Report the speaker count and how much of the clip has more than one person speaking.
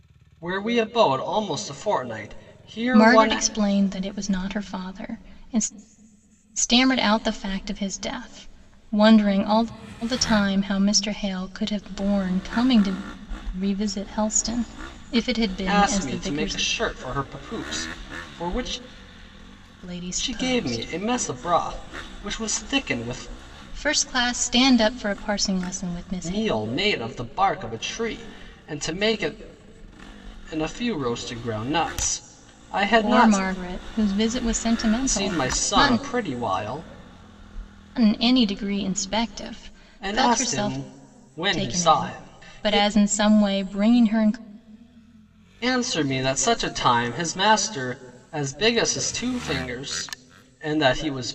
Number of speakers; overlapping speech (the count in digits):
2, about 12%